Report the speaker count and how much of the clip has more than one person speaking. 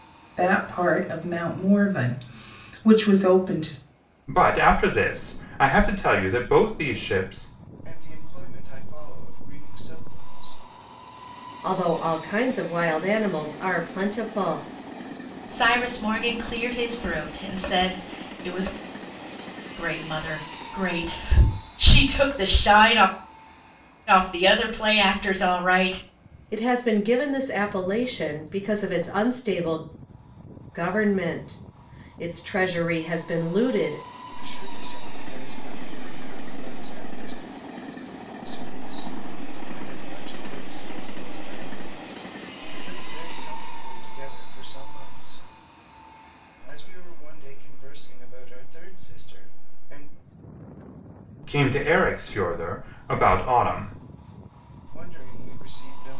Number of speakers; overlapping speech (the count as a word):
five, no overlap